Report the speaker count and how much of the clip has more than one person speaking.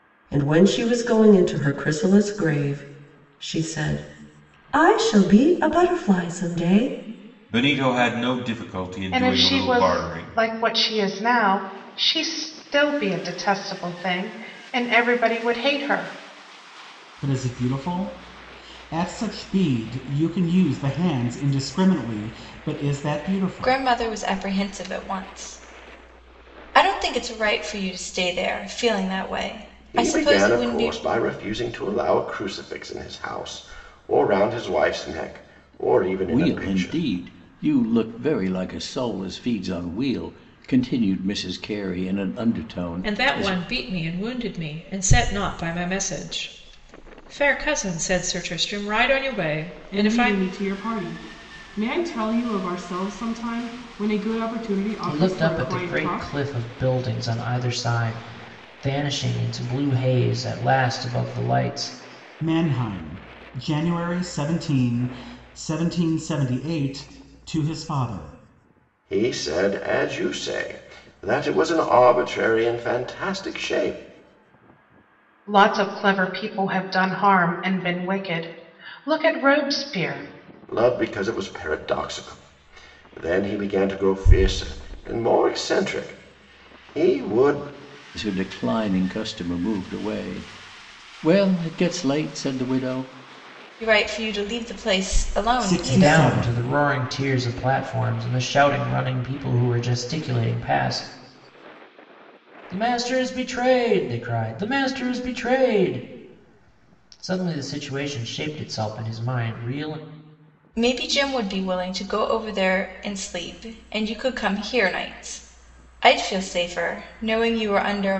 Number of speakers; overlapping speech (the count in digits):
10, about 6%